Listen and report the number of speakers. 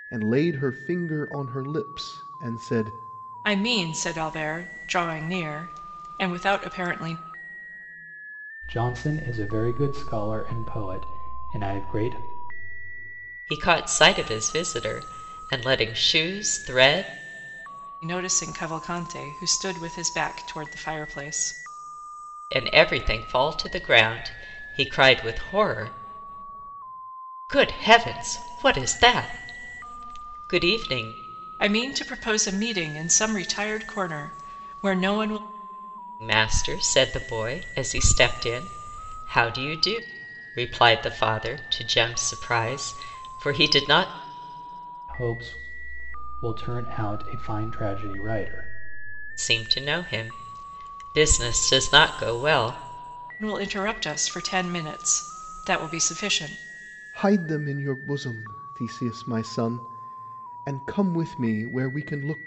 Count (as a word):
four